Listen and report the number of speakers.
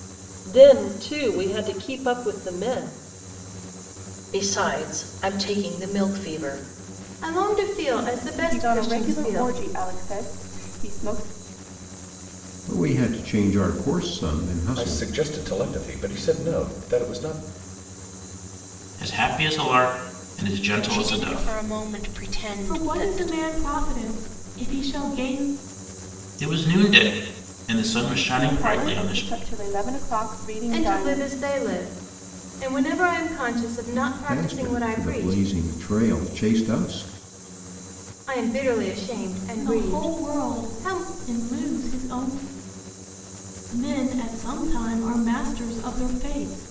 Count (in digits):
9